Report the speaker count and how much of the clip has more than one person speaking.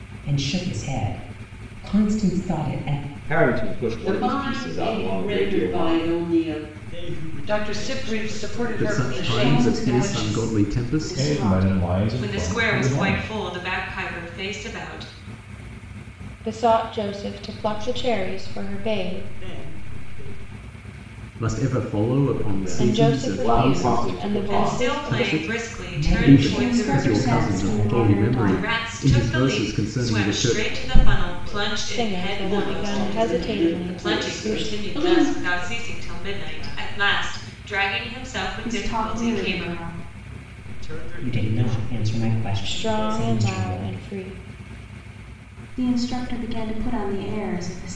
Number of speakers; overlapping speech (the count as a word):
ten, about 60%